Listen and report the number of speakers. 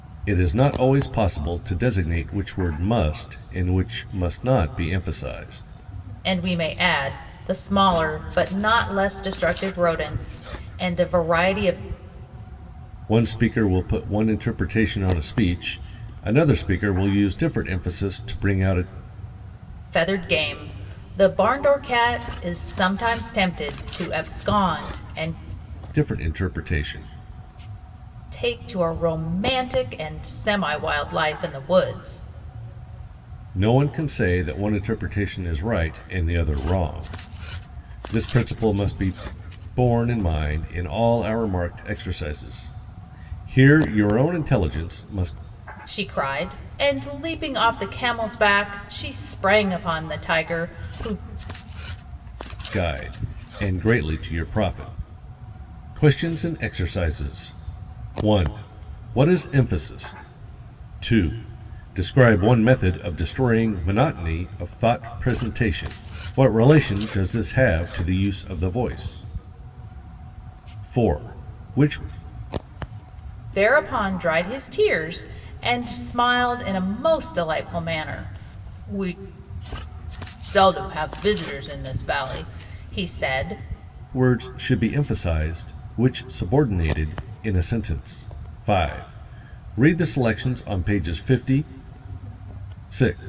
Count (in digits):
2